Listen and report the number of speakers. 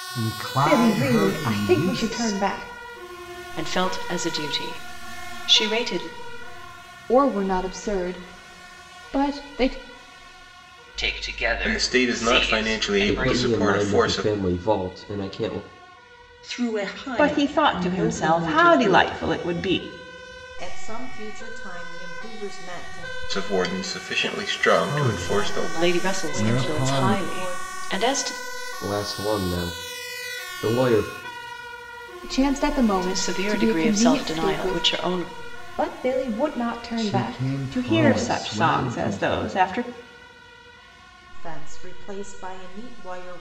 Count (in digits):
10